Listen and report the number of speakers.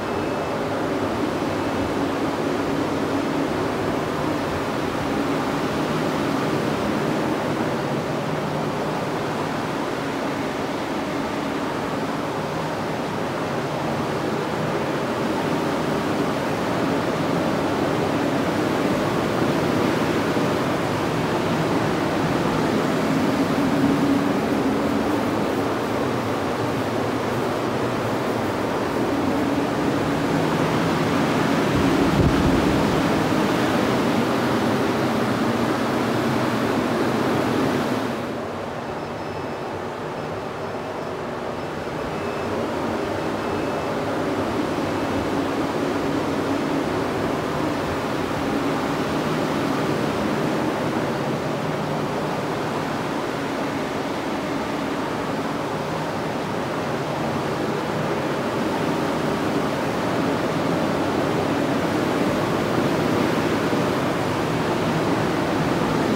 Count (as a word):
zero